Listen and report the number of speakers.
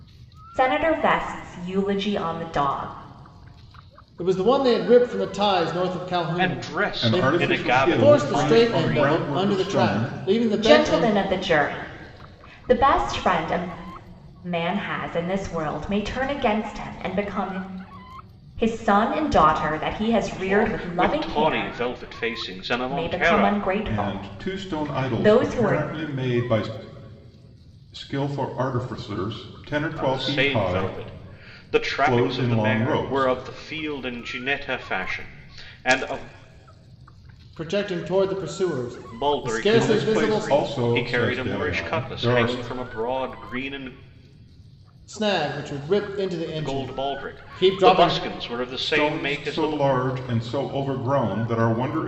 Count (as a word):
four